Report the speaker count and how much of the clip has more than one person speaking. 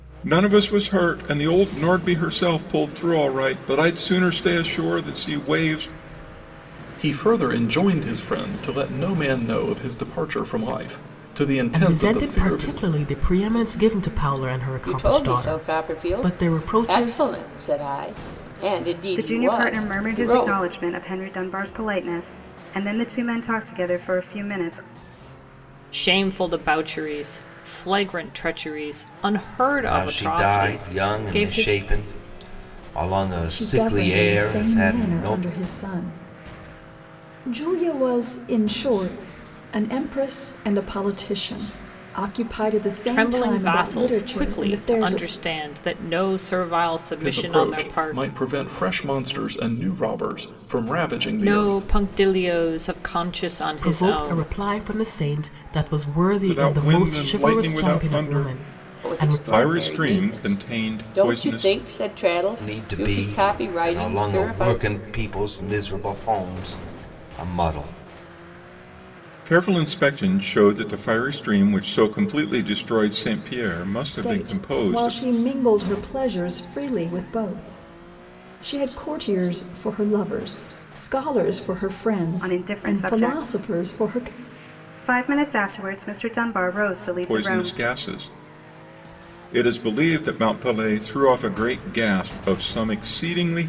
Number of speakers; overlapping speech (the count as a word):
eight, about 27%